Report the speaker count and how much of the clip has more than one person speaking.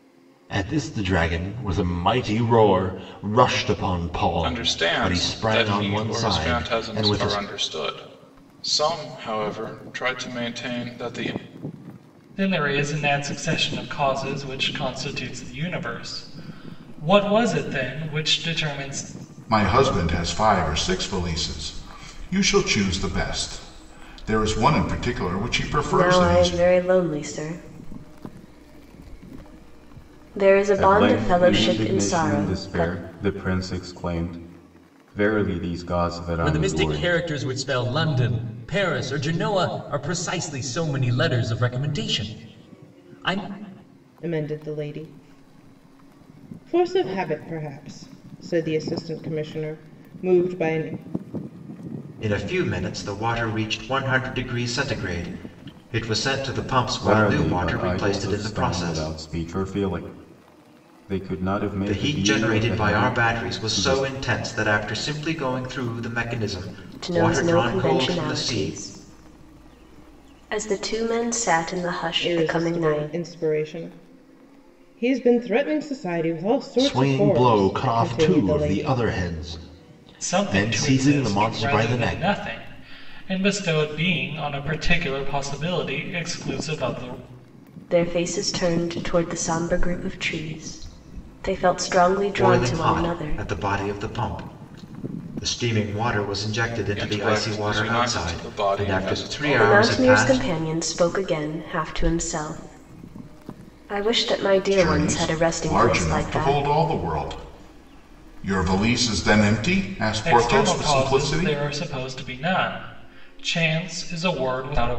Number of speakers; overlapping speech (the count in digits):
9, about 23%